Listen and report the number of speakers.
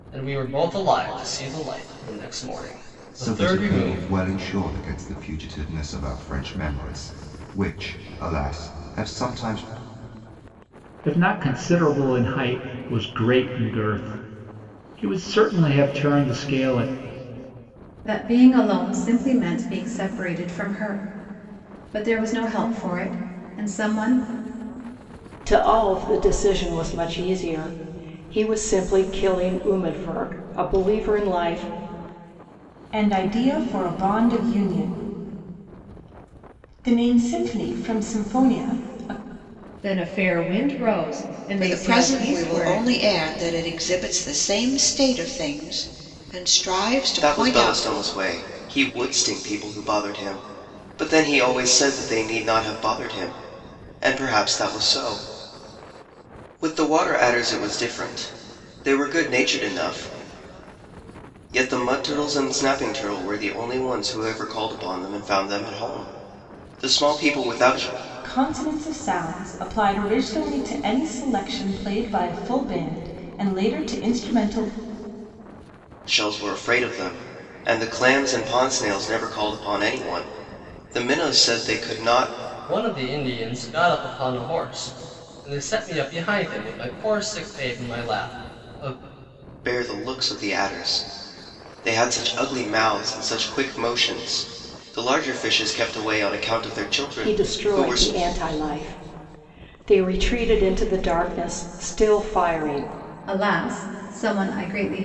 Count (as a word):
nine